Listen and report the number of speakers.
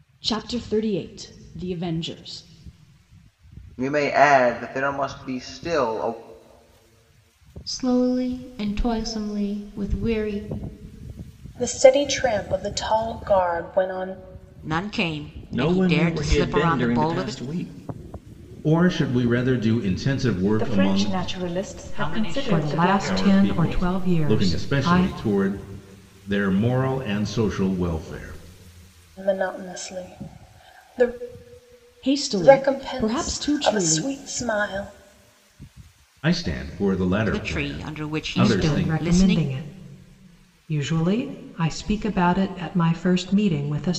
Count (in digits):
10